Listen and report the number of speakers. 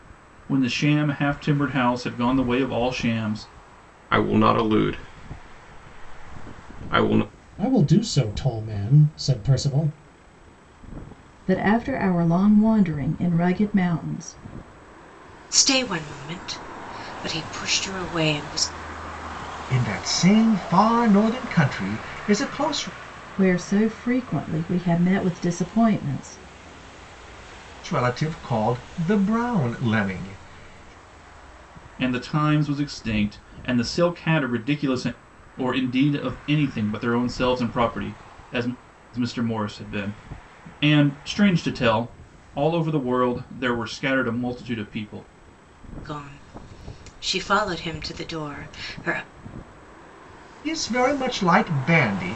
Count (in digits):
6